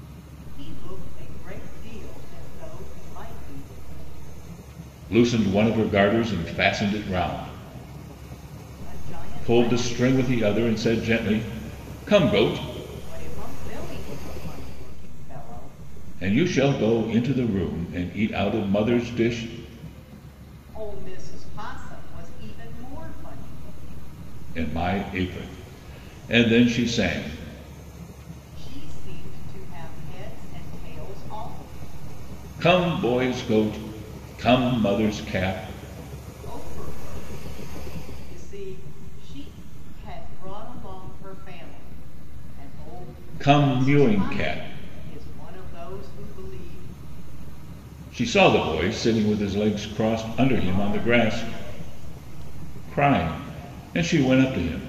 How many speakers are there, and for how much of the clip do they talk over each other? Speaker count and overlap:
2, about 5%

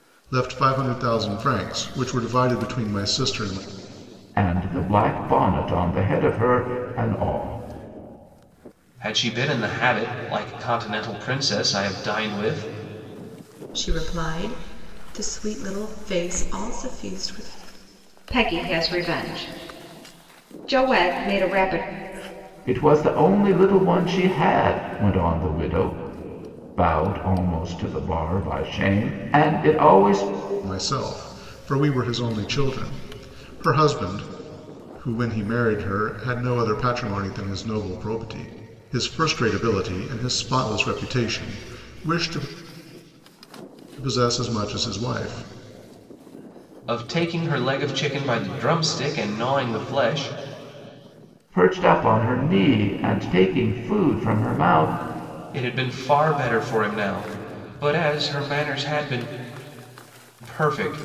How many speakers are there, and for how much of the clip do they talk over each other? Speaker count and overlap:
5, no overlap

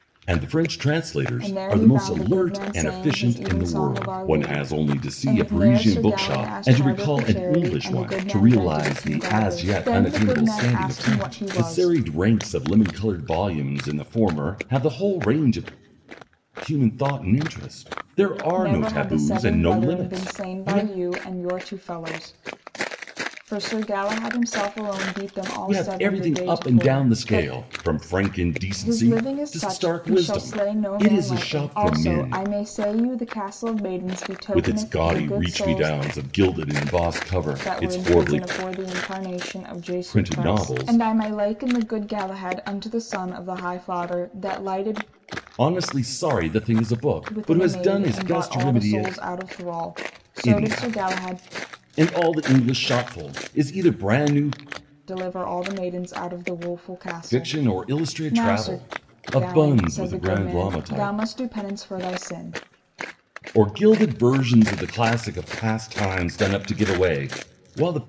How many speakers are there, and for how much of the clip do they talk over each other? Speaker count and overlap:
2, about 41%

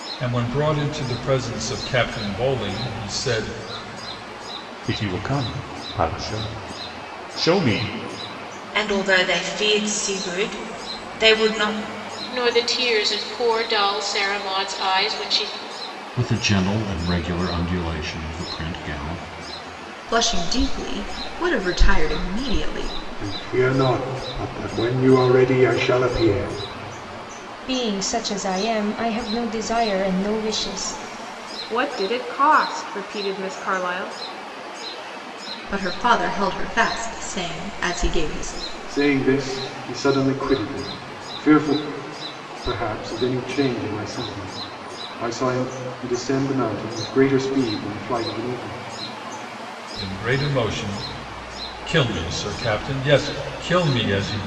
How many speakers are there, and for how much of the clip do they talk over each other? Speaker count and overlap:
9, no overlap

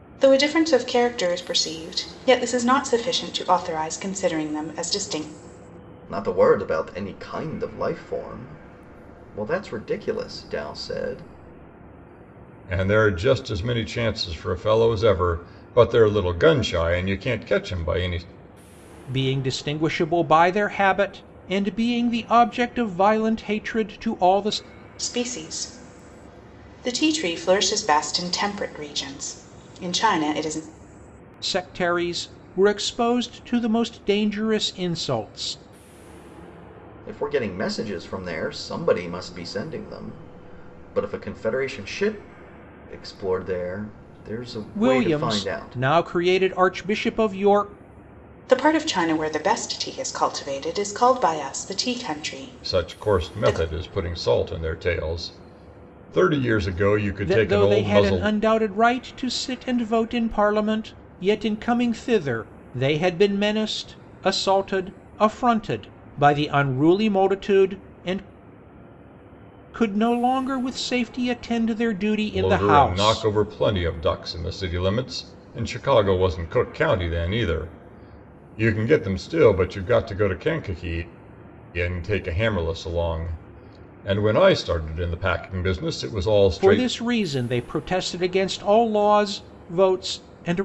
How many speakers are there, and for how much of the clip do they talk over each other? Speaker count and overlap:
4, about 5%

